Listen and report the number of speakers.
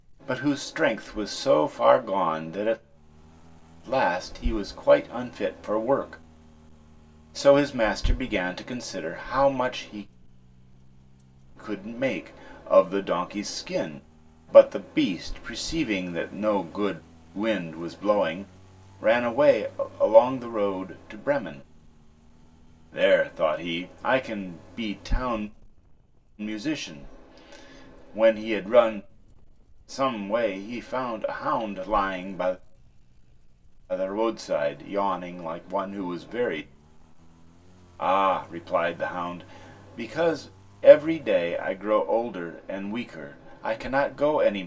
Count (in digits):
1